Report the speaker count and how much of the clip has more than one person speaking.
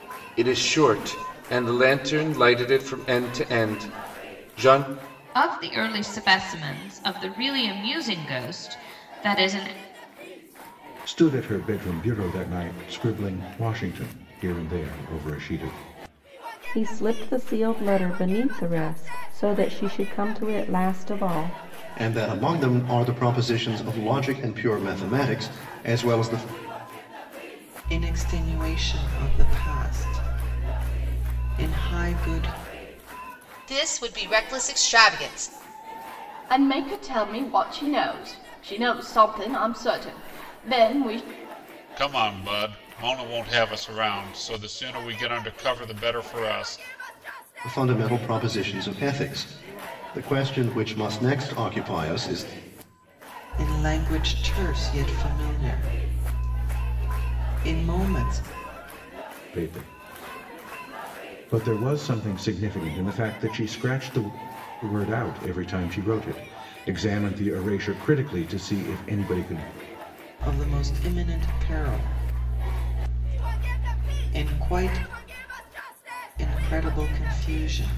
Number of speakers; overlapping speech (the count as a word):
nine, no overlap